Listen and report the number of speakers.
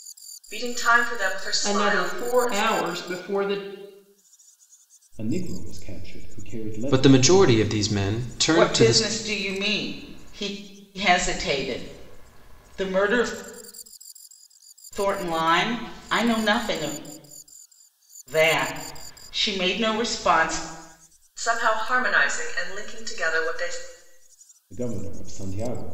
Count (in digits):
5